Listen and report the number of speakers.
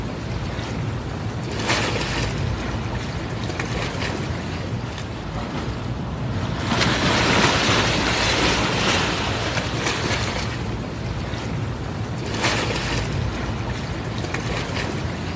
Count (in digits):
0